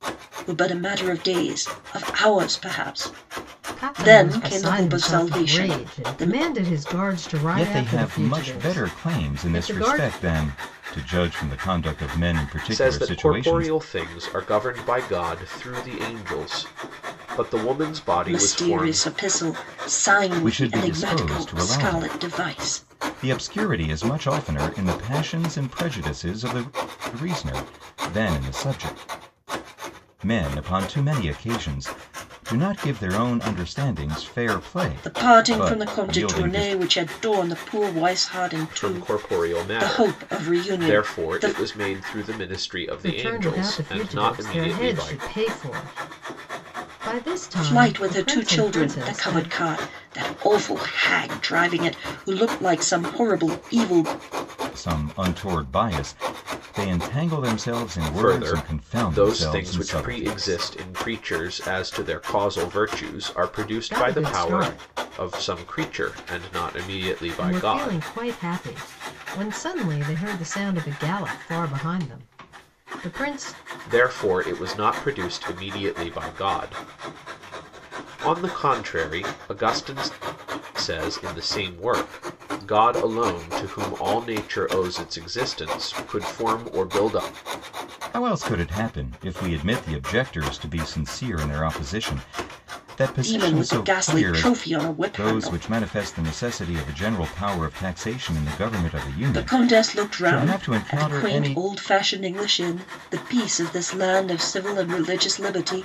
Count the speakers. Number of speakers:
4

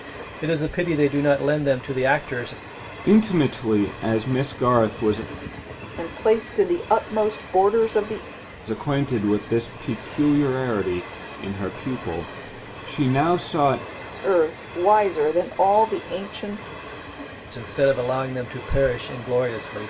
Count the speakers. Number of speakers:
3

